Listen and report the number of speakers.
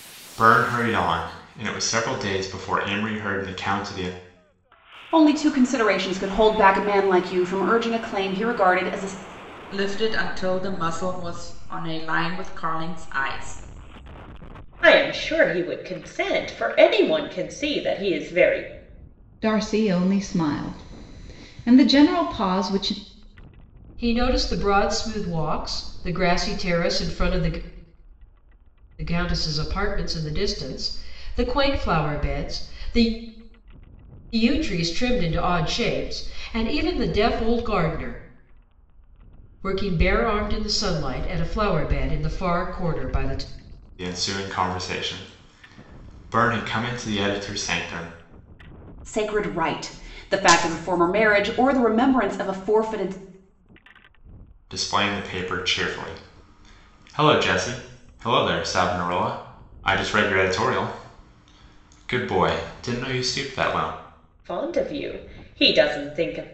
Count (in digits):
6